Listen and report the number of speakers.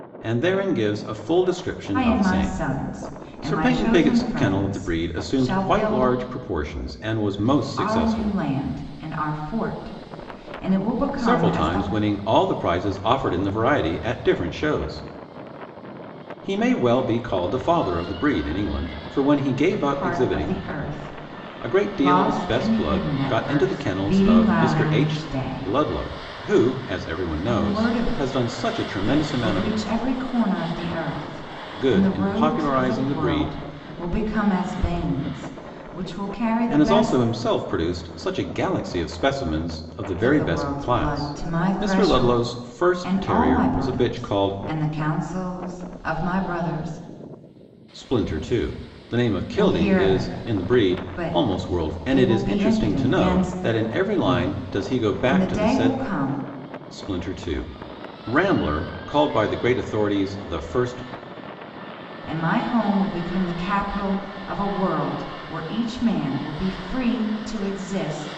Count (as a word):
two